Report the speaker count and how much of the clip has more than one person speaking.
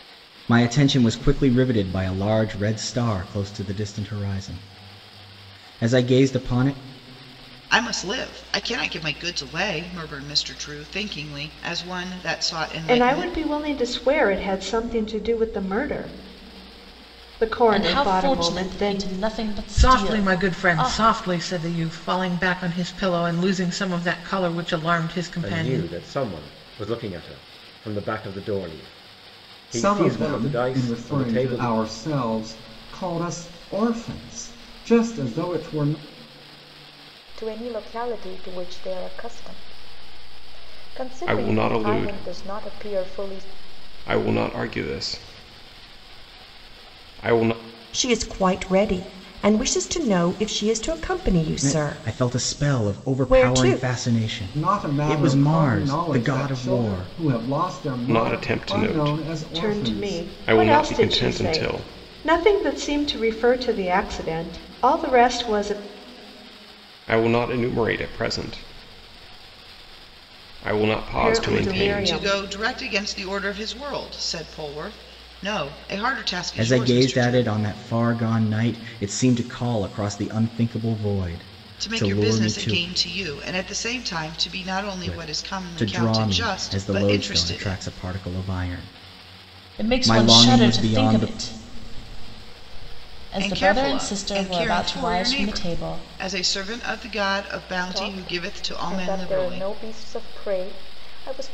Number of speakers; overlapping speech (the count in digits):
10, about 28%